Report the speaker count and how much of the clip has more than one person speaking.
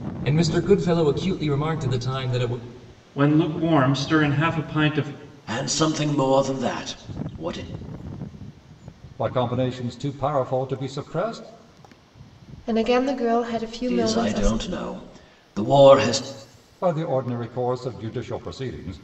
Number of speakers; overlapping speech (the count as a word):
five, about 3%